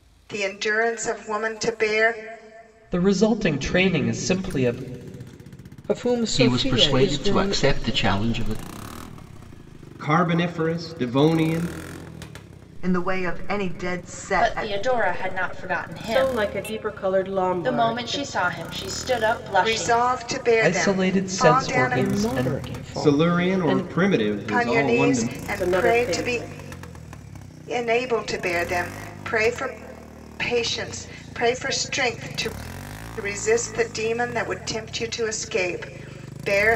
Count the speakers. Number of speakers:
8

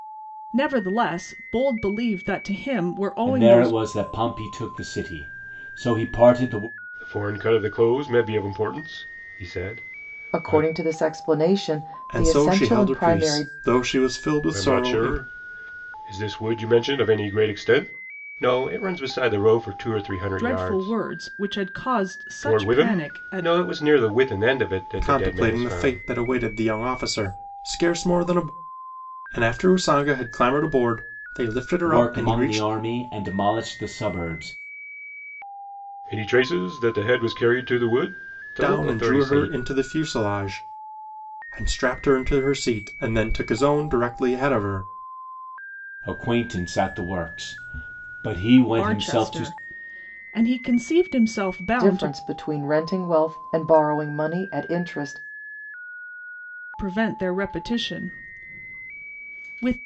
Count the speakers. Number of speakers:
5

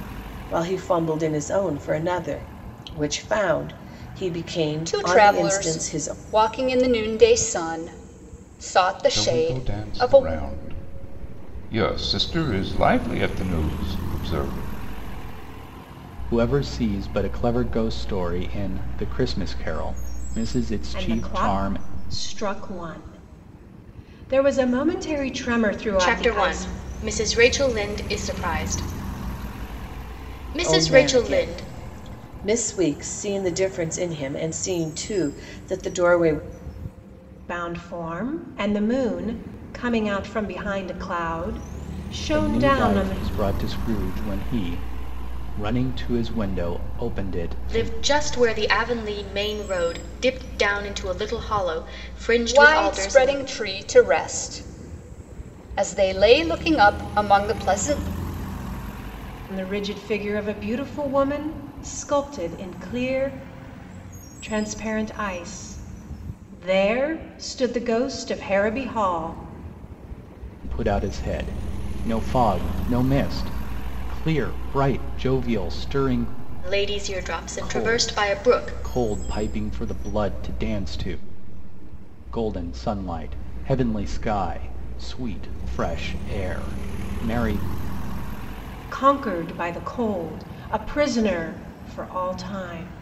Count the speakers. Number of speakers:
6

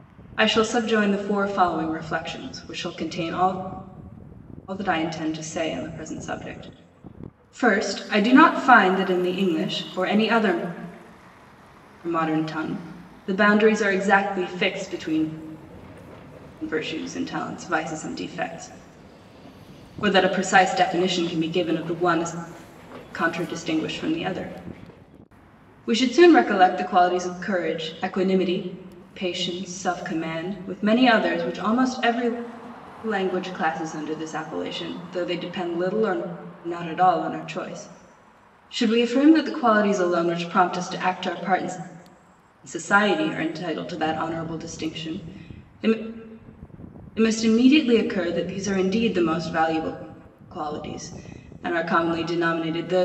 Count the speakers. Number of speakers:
1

